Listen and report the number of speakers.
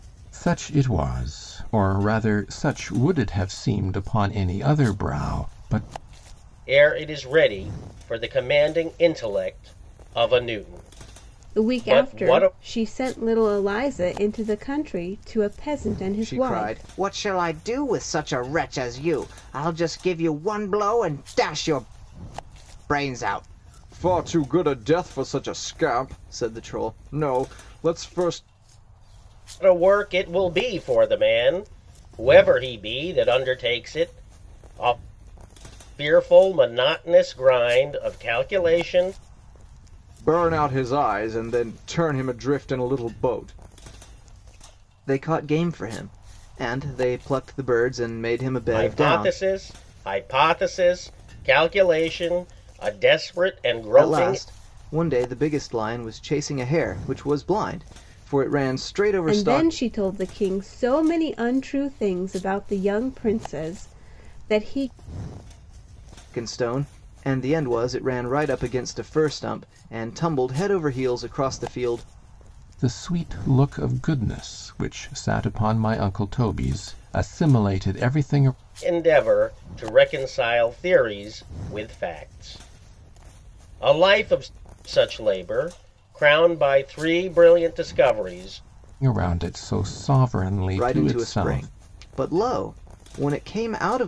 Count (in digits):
4